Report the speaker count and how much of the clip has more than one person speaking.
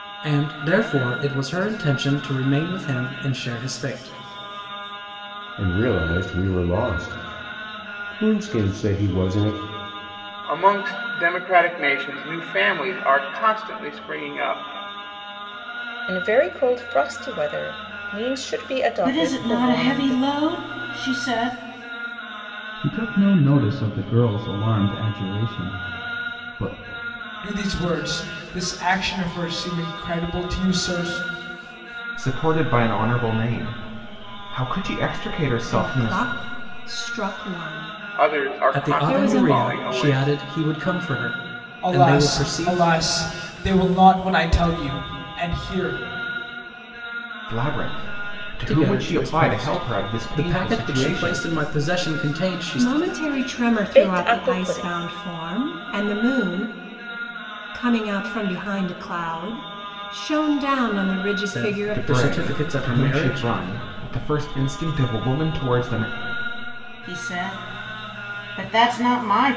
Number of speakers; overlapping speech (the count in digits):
9, about 19%